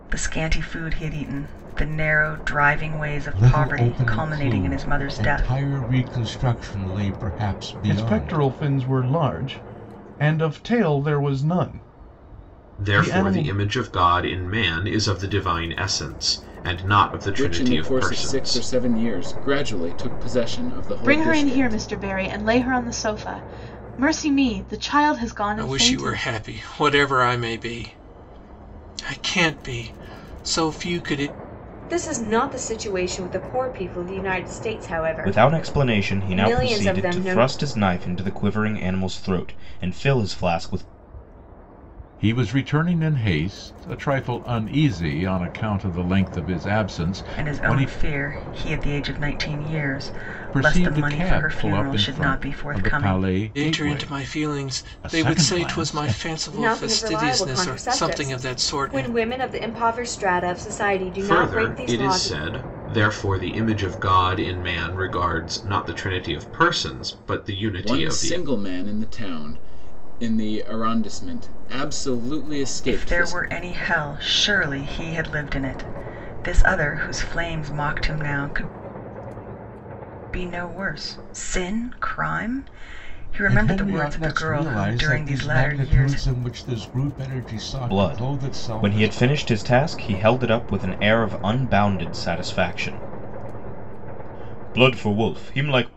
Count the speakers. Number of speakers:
10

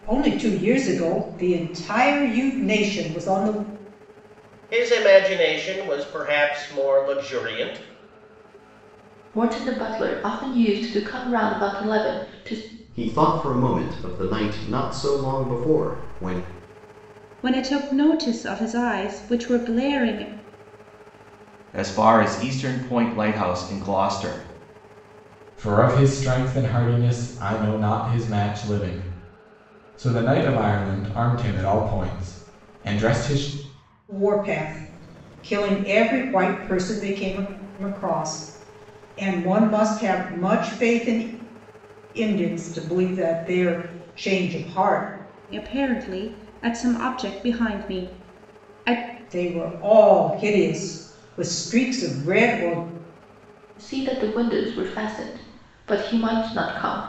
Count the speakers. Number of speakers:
7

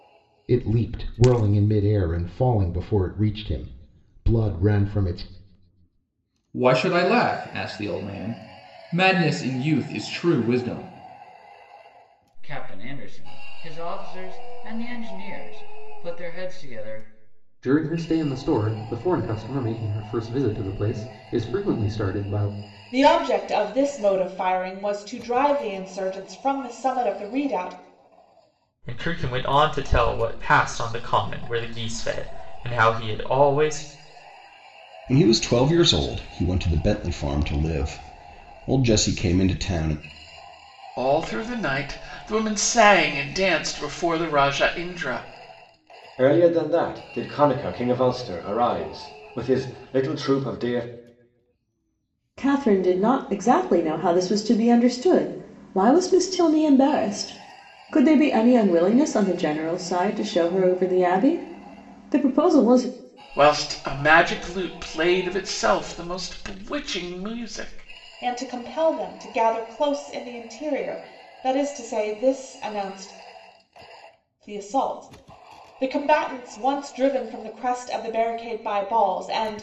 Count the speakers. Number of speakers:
10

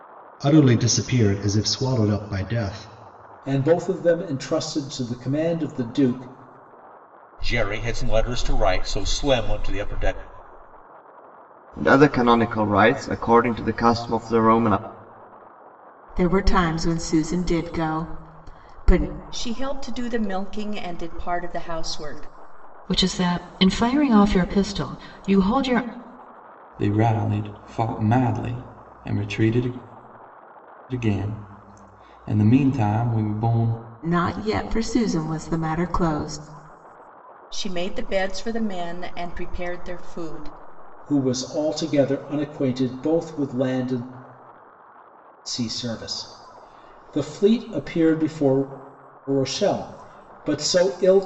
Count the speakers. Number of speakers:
8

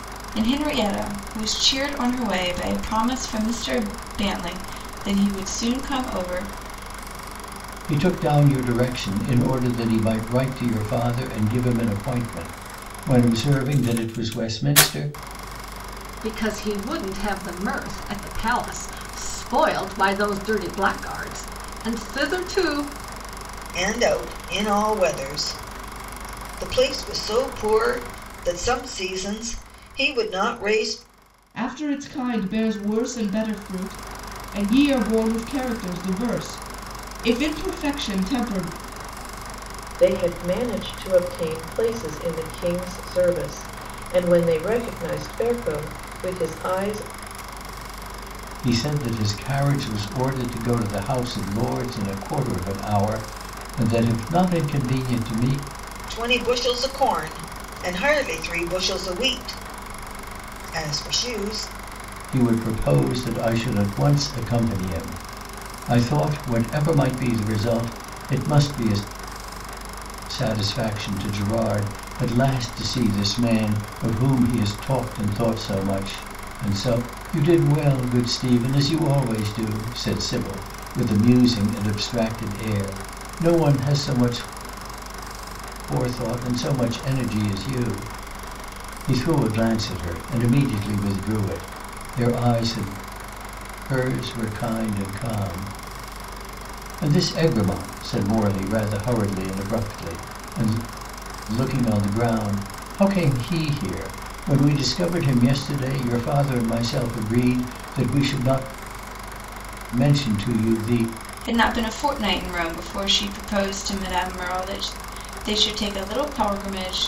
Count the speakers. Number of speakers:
6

